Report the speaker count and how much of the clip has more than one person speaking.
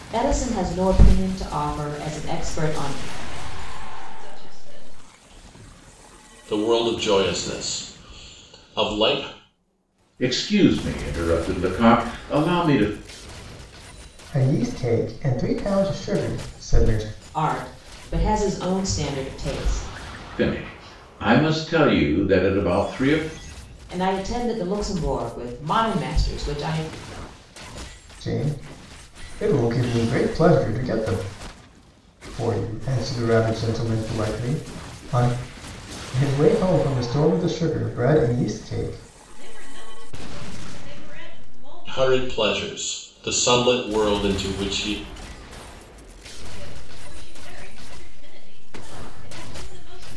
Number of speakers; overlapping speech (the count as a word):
five, about 3%